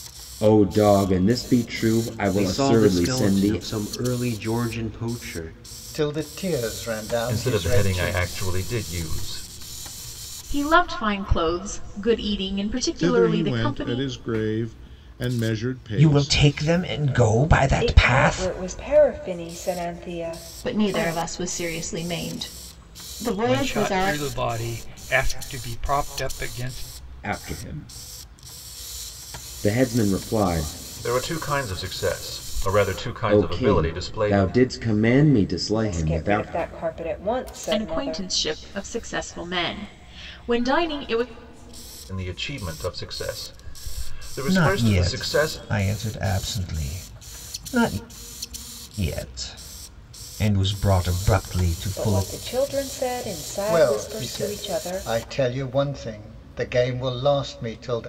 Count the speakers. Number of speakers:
ten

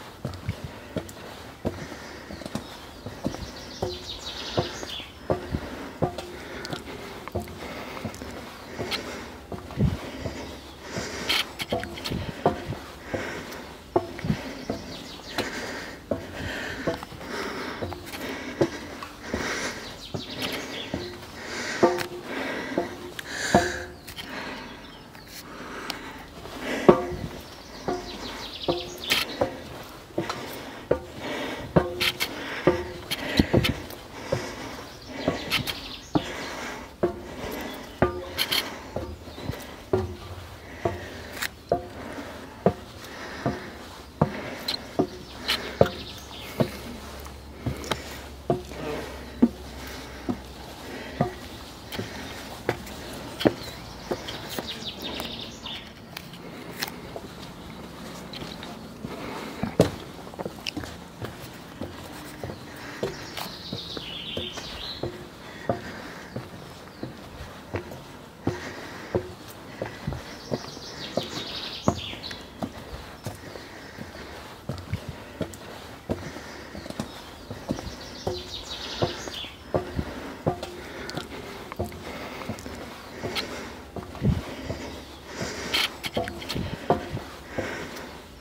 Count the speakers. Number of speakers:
zero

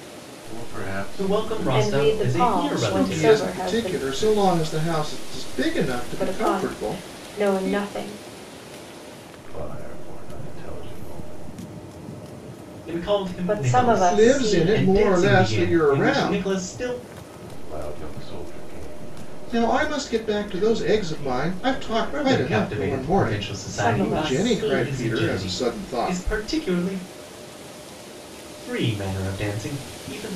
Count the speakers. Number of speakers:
four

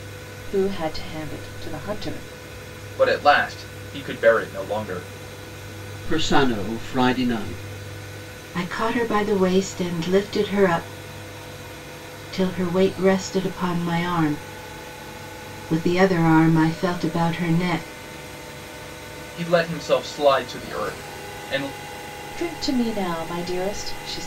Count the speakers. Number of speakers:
four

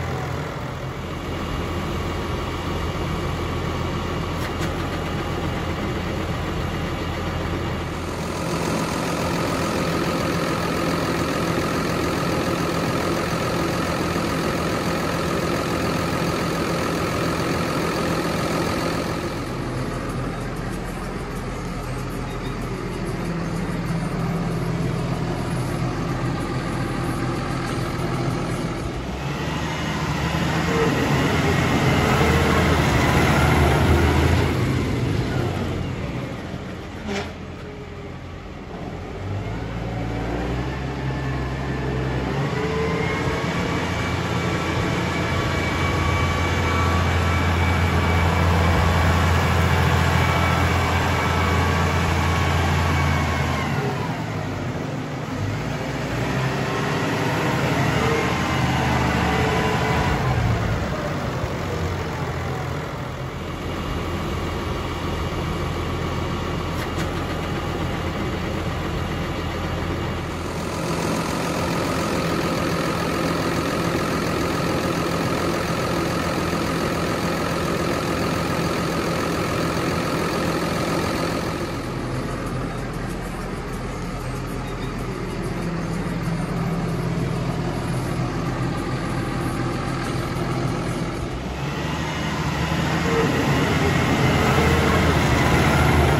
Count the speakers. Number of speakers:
zero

